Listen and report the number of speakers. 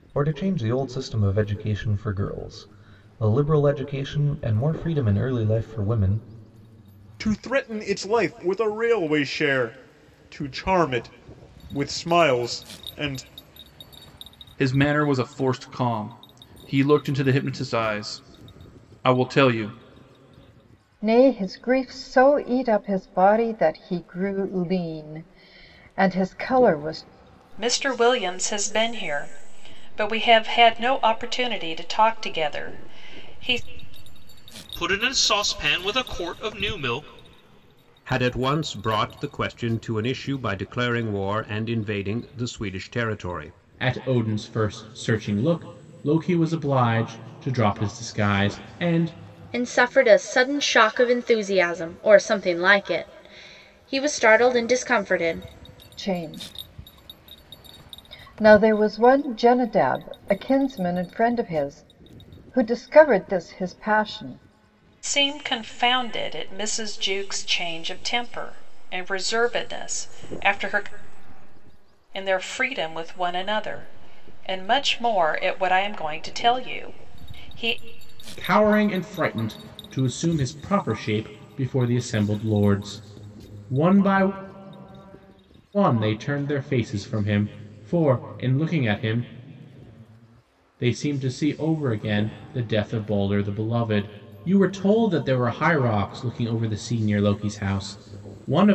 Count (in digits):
9